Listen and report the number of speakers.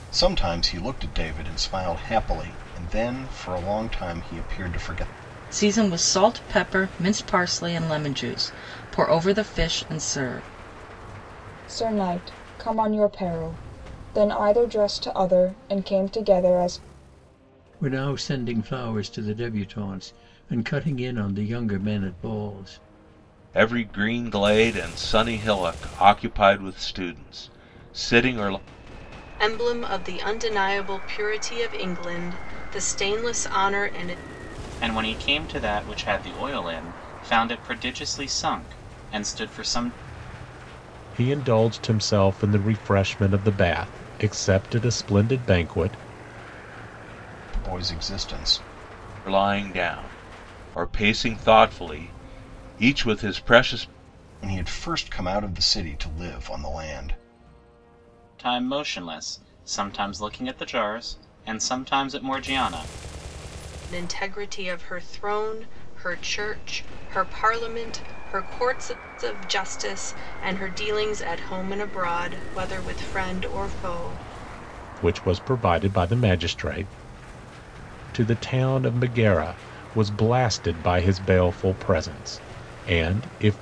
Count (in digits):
8